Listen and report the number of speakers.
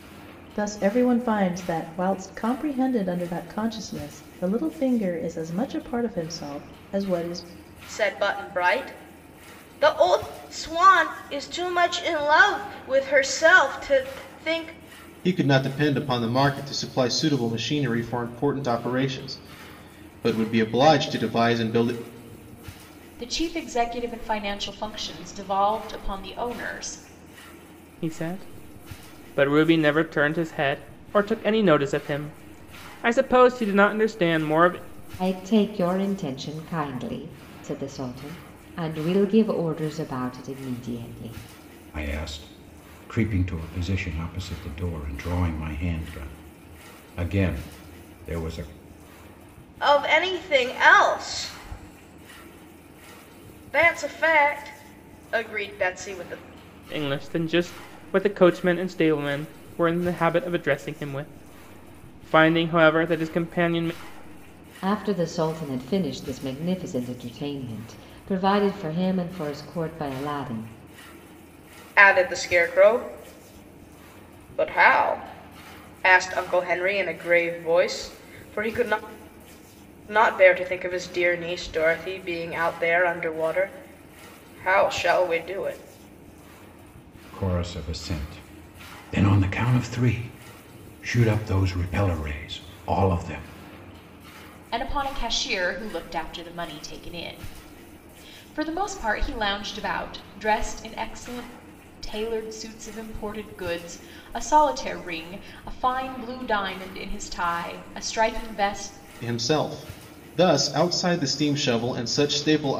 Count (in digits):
7